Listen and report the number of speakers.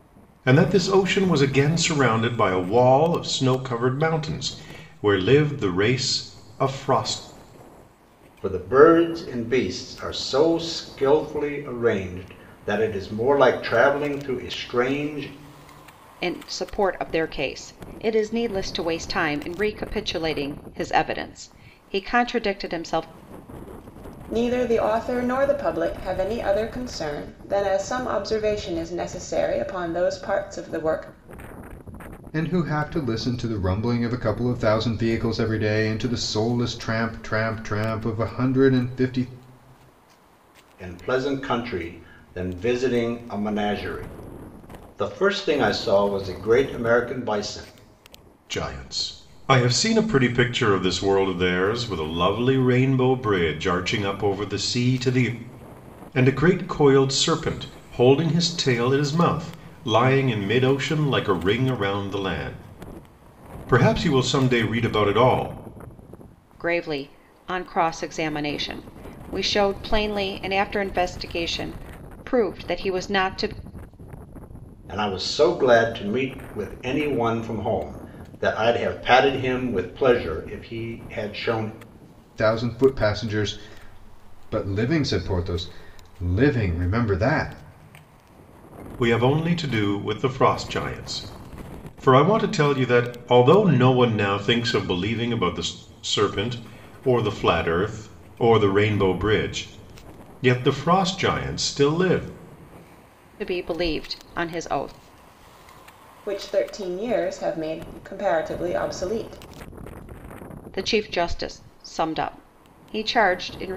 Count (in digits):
5